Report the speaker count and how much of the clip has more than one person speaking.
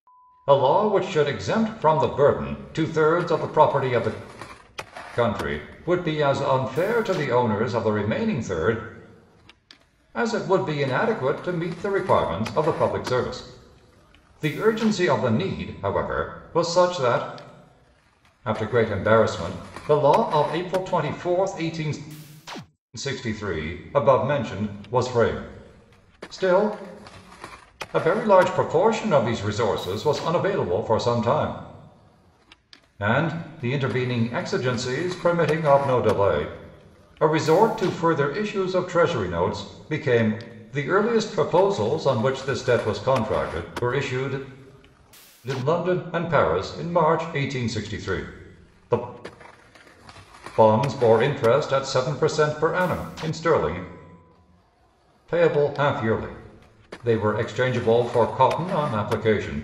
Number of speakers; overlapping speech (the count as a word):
one, no overlap